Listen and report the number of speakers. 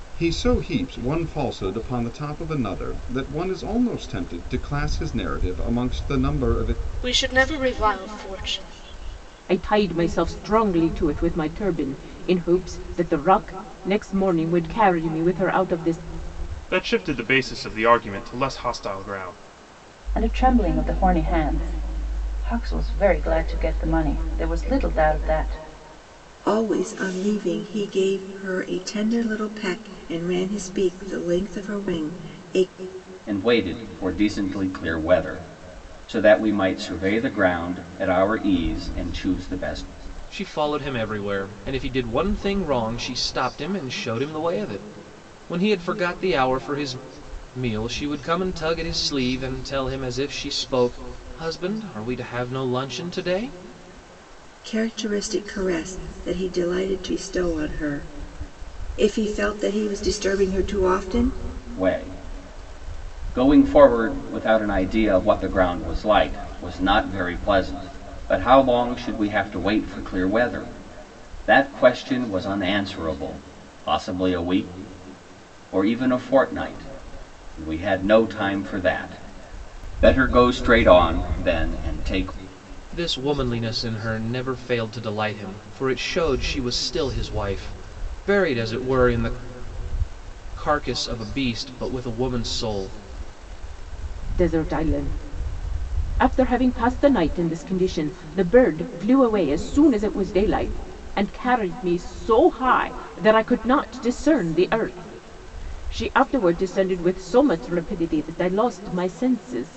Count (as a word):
eight